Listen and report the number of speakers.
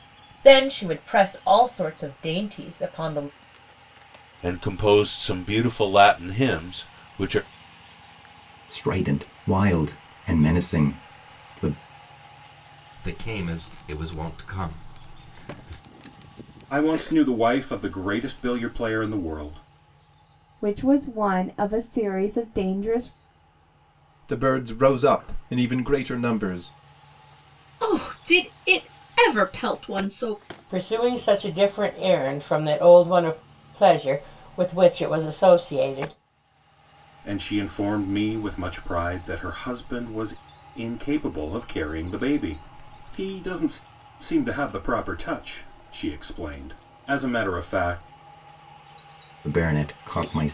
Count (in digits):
9